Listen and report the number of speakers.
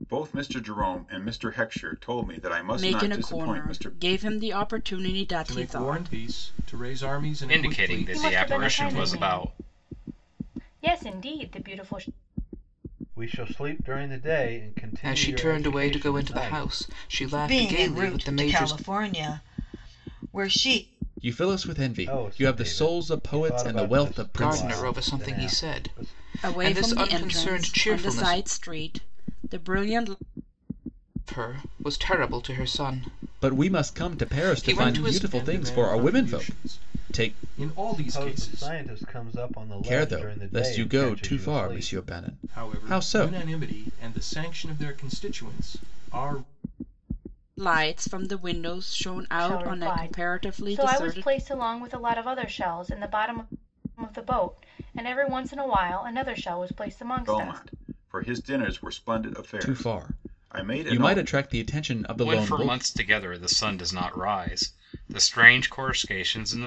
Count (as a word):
nine